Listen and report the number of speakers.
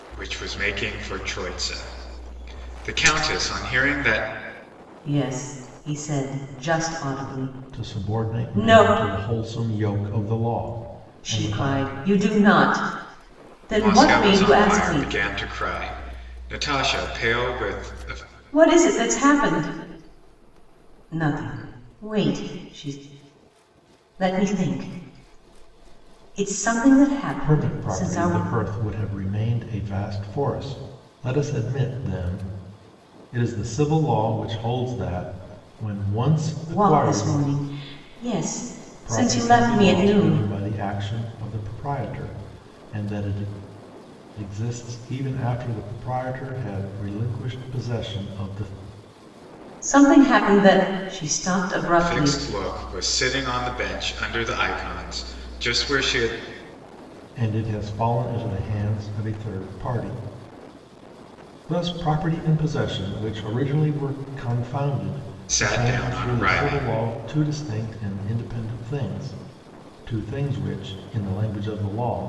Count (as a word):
three